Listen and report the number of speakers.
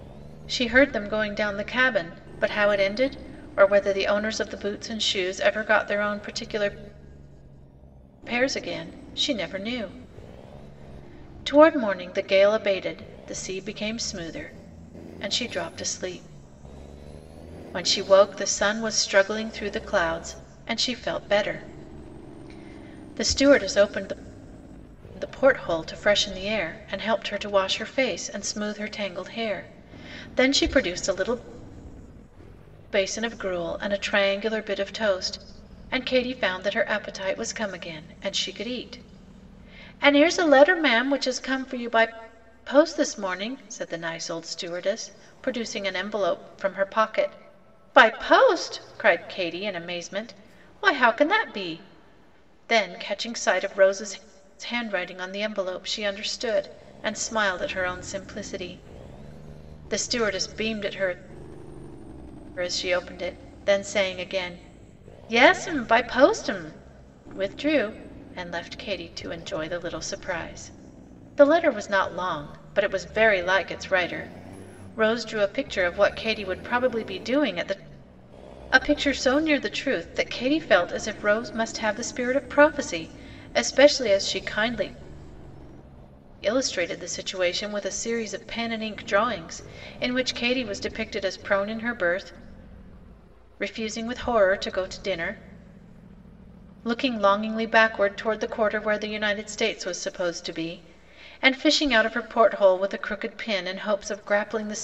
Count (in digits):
1